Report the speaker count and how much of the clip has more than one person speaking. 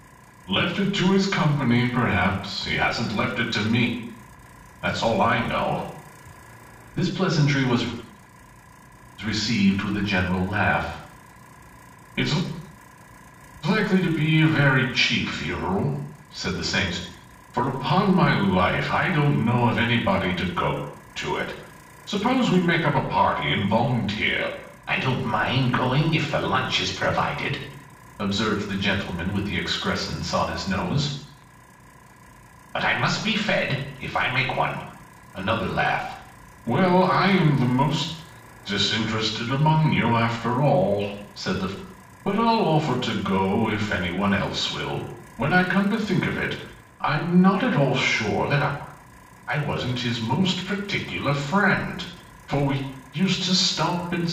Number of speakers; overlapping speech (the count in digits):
1, no overlap